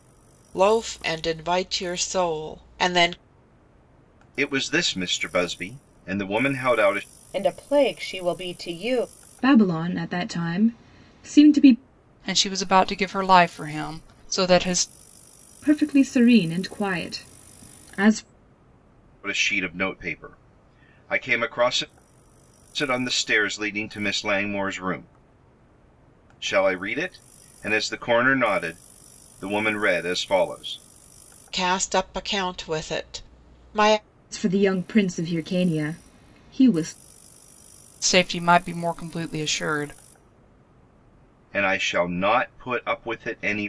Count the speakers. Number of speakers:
five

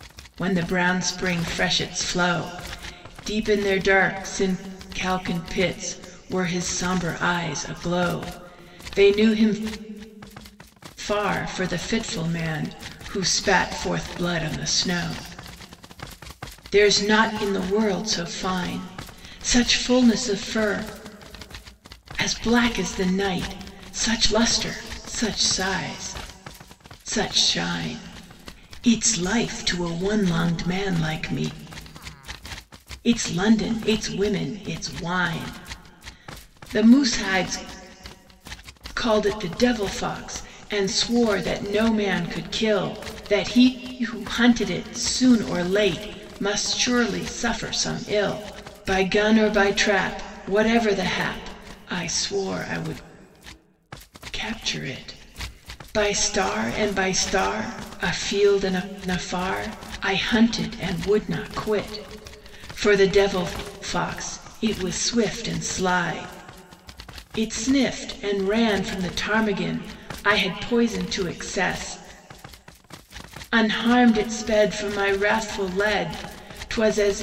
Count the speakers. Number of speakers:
one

